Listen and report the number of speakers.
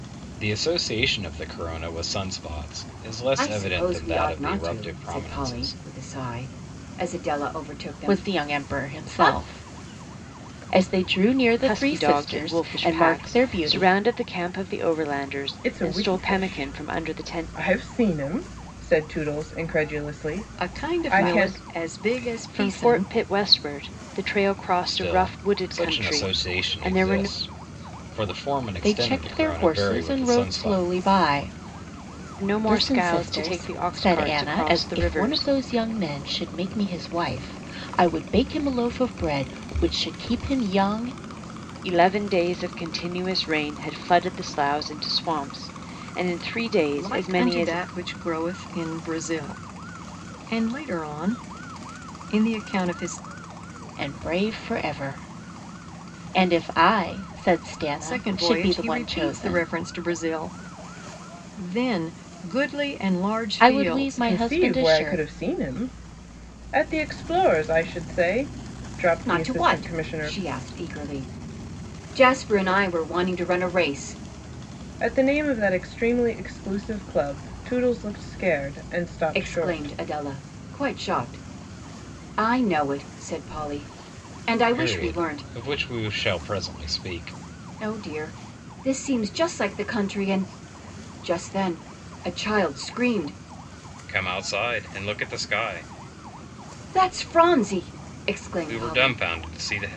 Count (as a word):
six